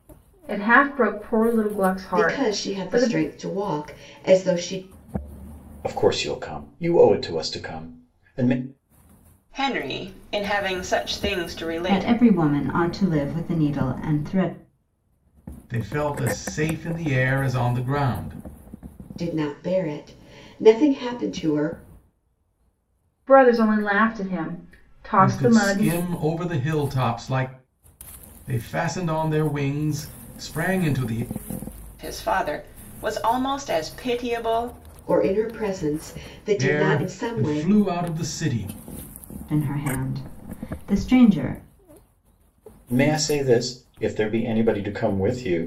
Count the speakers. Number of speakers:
6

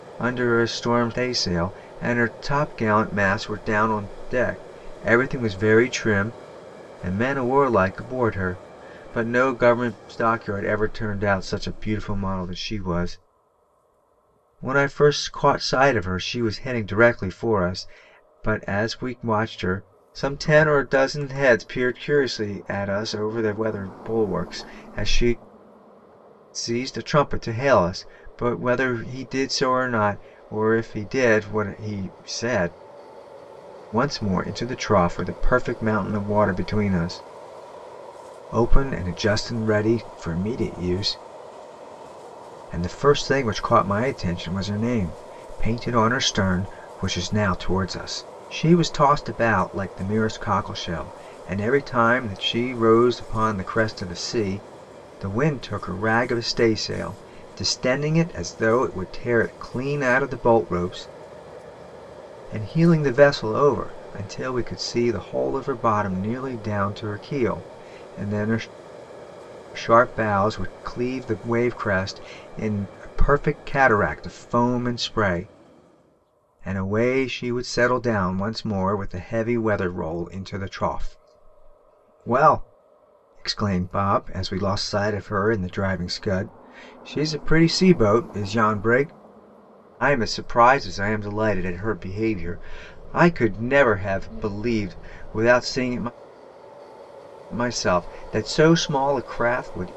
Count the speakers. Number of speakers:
1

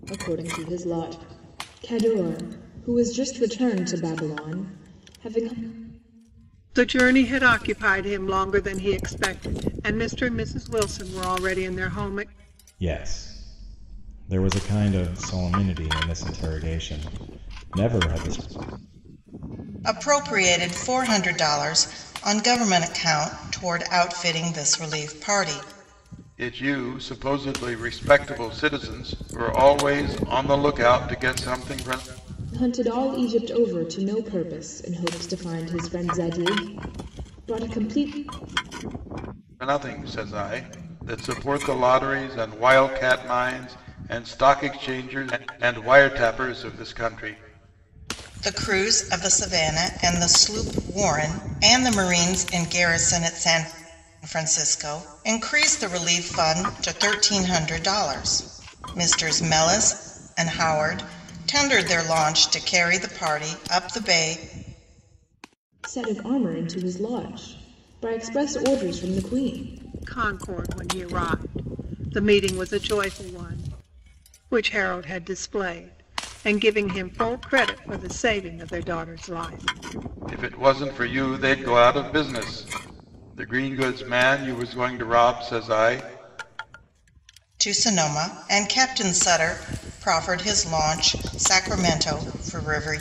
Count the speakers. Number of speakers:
5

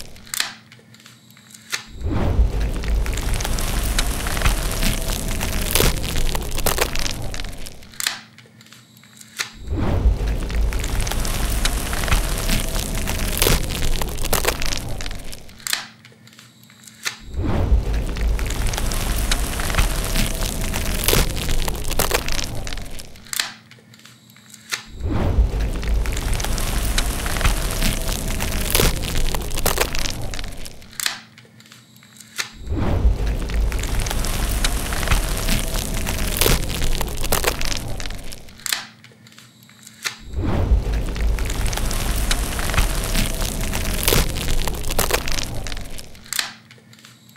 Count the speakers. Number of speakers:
0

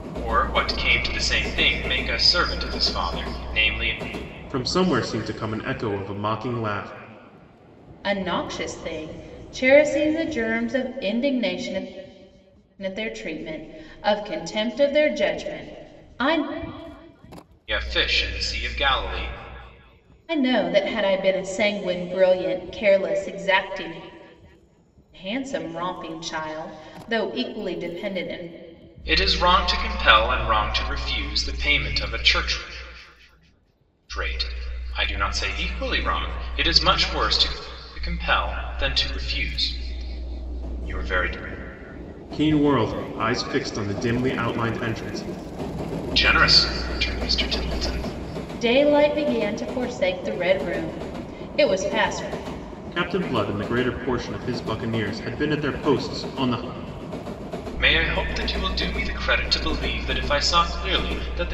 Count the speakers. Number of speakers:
3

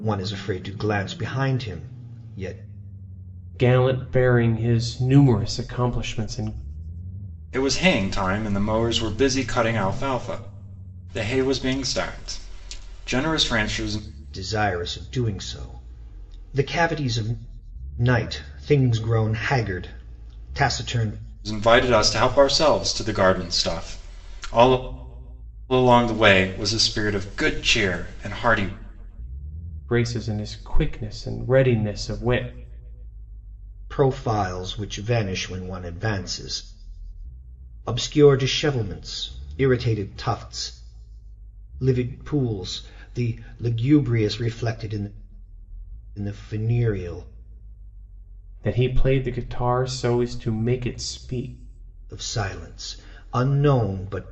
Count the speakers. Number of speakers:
3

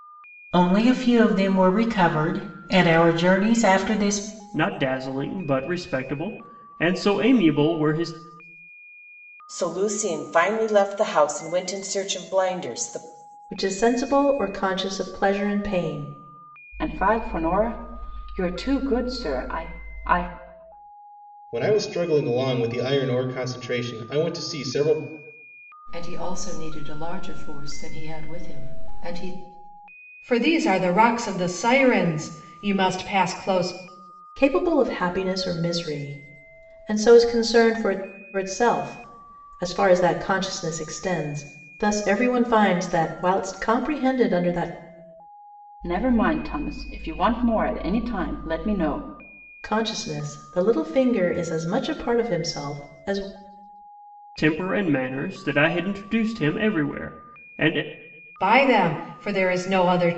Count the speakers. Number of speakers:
8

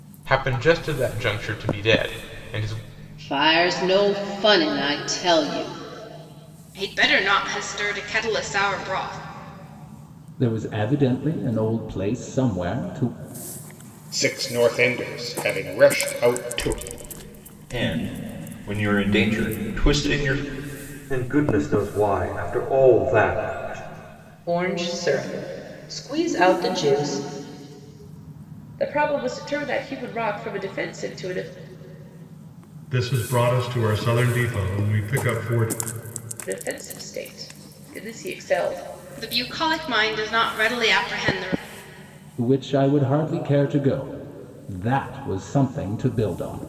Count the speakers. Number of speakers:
10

